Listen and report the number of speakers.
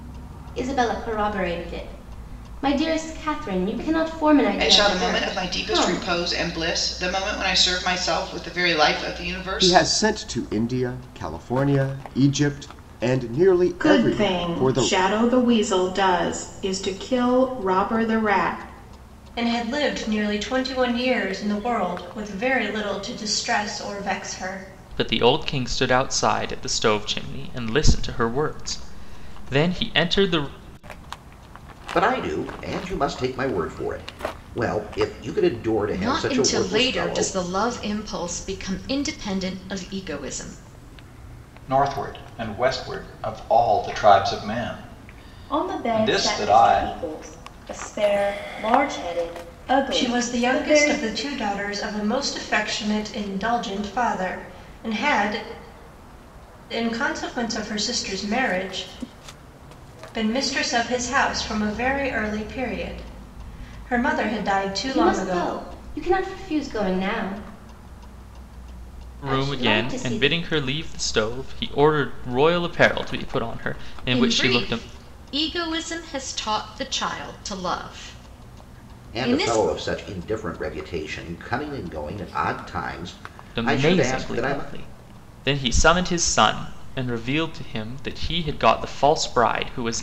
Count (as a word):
ten